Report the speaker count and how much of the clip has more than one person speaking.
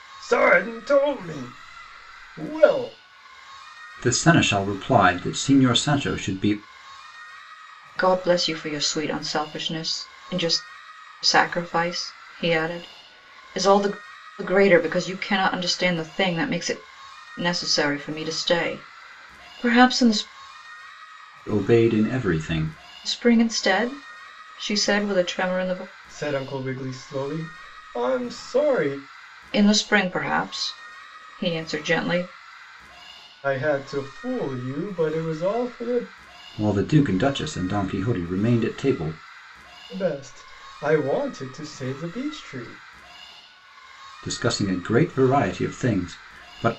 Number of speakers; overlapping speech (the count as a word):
three, no overlap